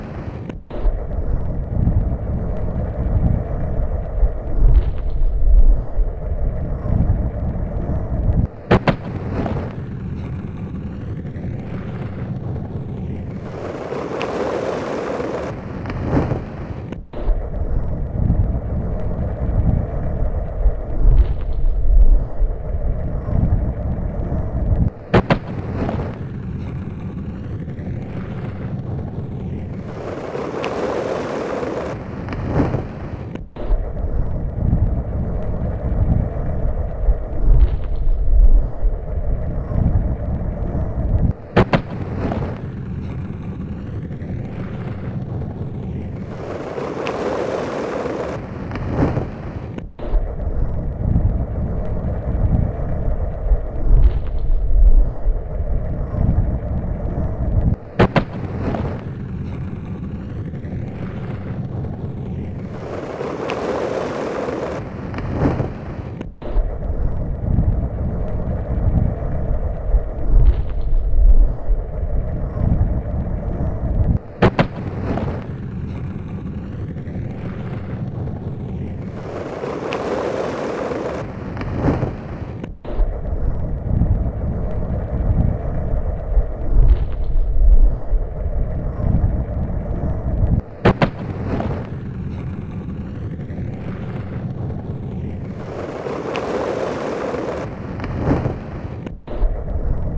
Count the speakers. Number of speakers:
0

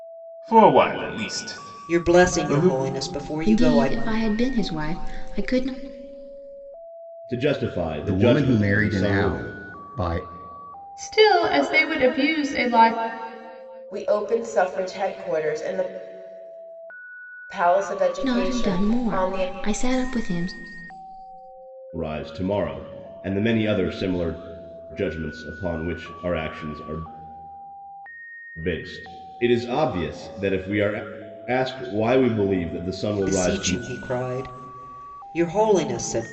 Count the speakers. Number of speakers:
7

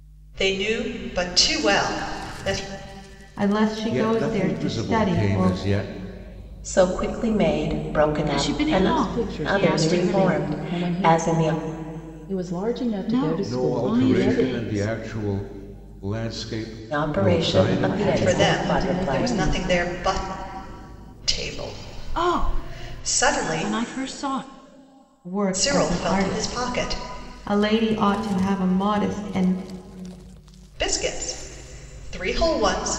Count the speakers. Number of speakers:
6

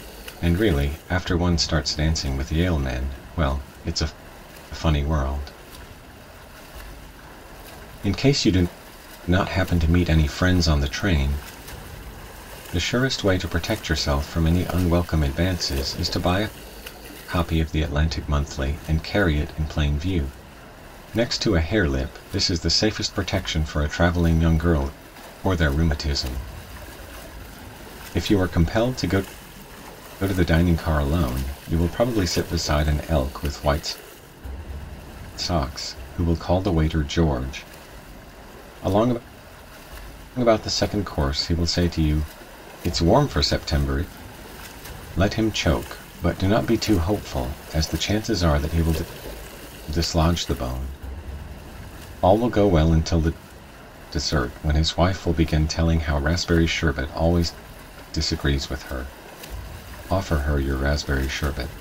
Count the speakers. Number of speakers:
1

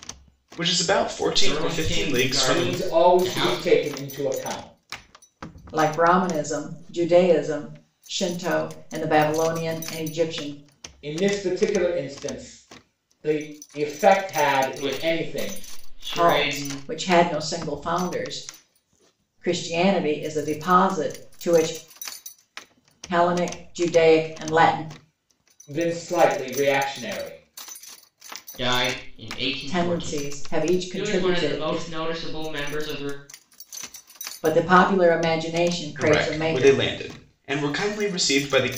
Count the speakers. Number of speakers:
4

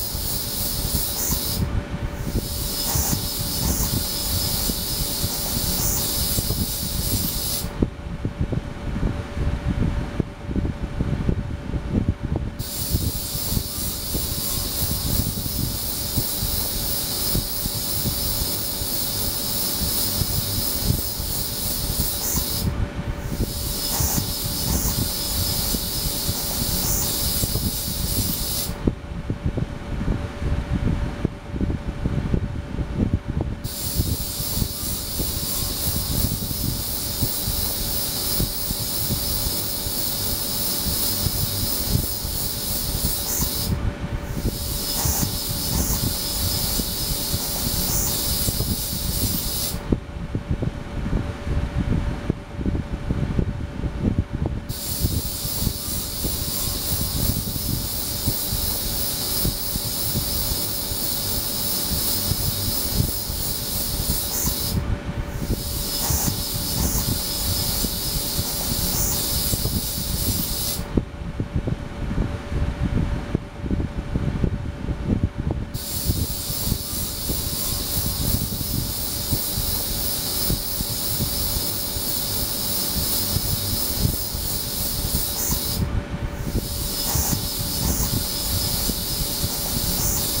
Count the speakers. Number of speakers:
0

